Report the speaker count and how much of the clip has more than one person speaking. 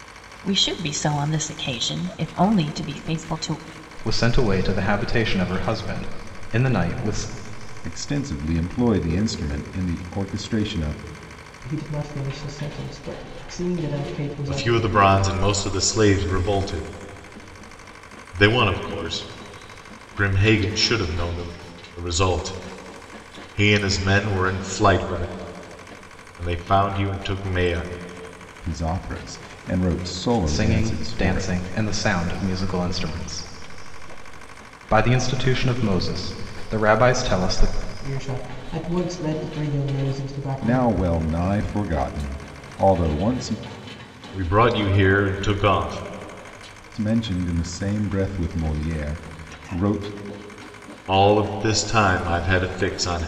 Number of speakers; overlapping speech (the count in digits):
5, about 4%